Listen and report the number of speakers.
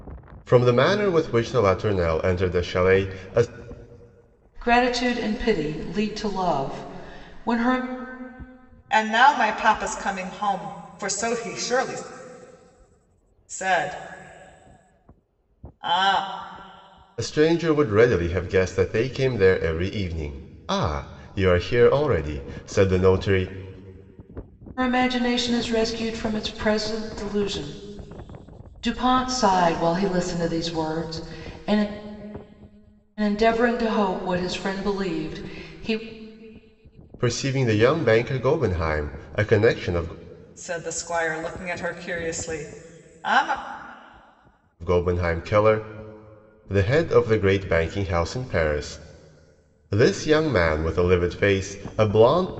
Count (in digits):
3